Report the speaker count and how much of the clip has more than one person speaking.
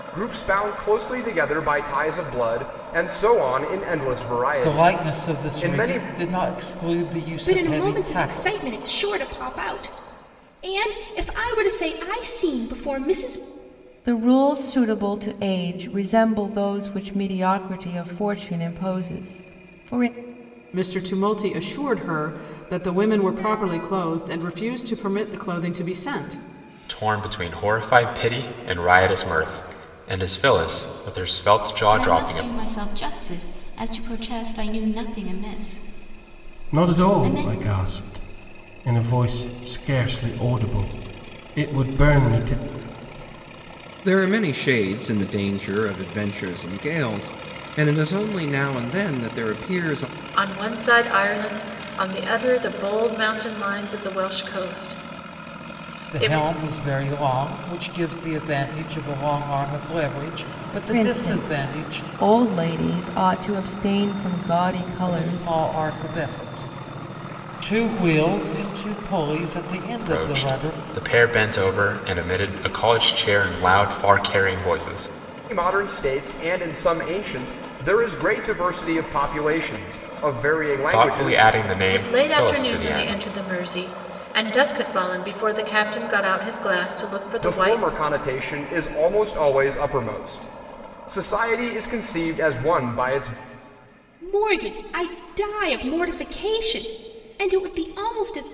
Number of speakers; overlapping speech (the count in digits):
10, about 10%